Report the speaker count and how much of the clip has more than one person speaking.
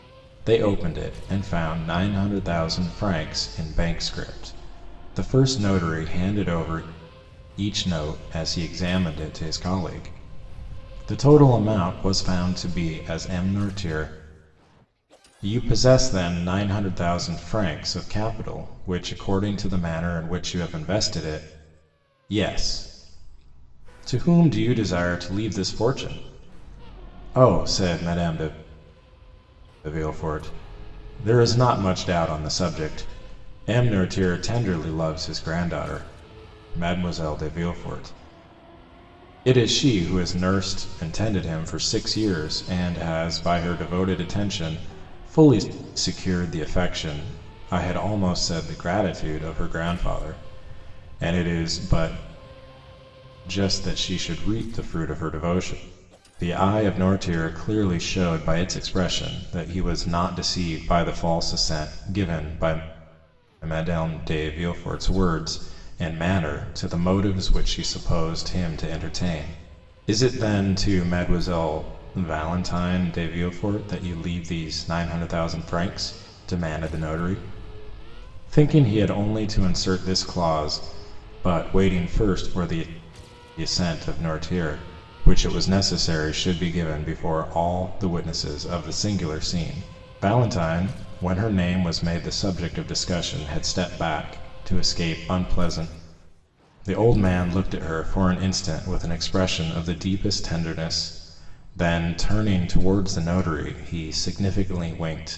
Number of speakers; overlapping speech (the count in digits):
1, no overlap